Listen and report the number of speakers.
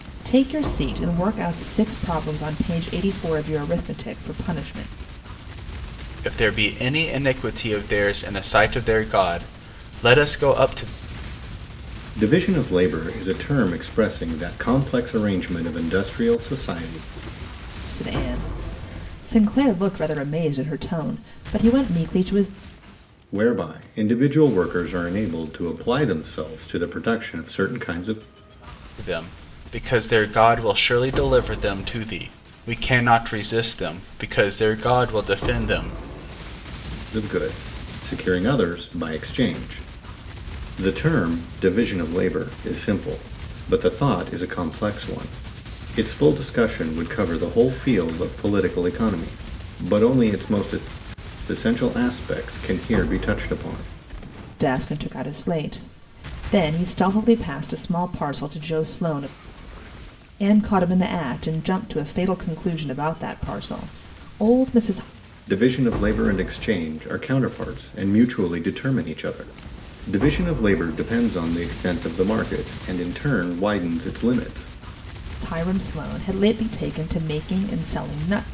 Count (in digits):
3